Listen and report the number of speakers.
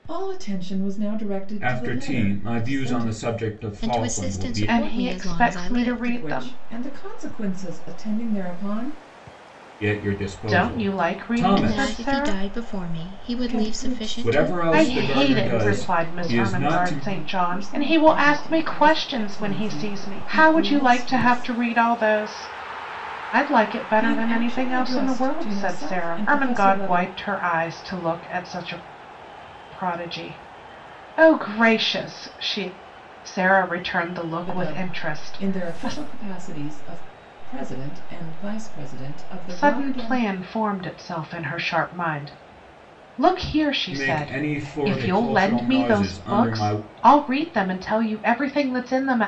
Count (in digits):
4